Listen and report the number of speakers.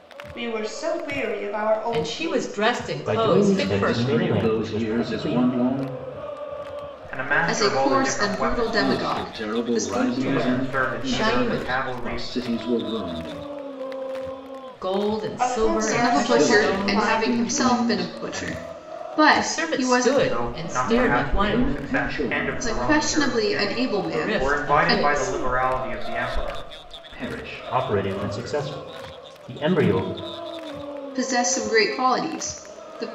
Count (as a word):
six